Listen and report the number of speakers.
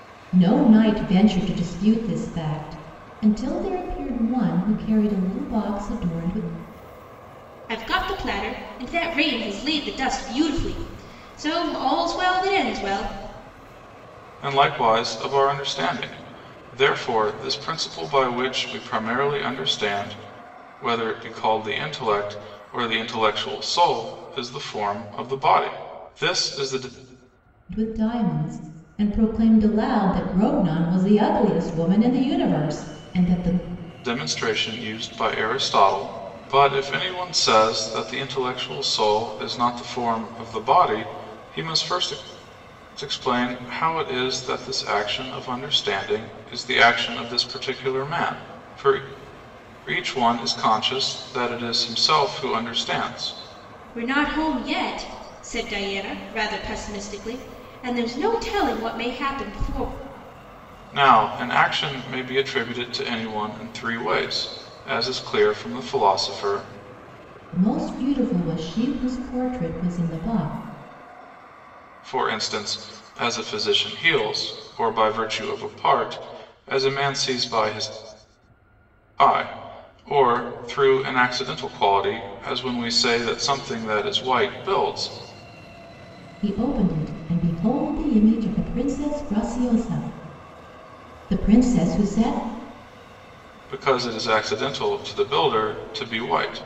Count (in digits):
3